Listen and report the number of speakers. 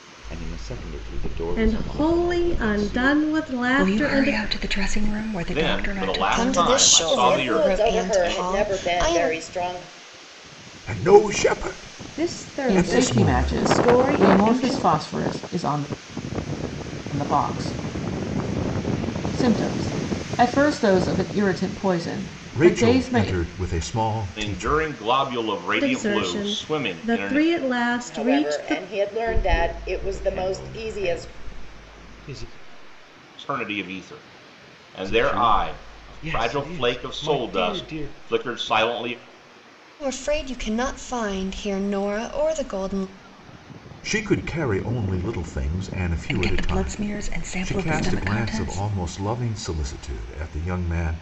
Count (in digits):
9